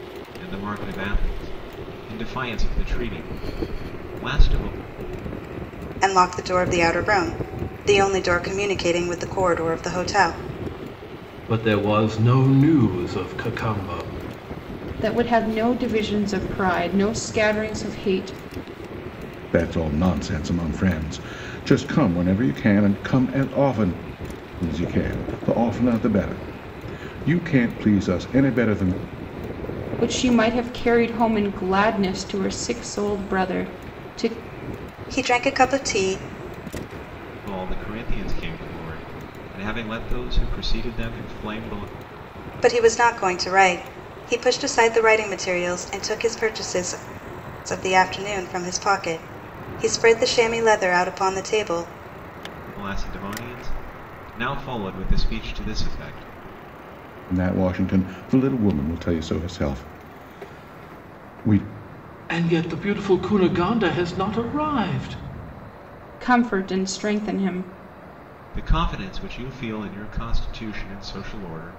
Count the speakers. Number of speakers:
five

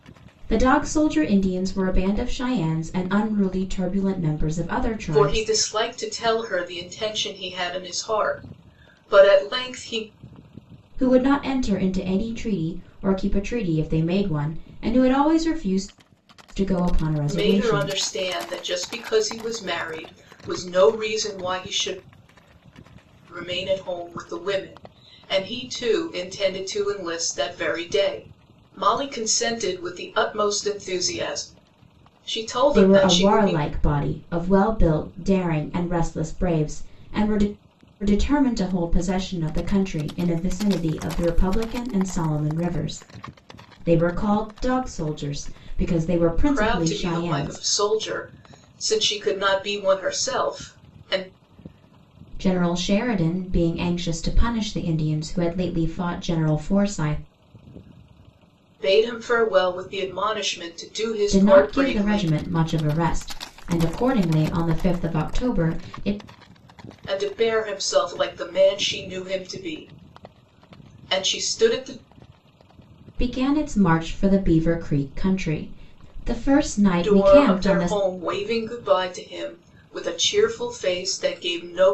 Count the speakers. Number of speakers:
two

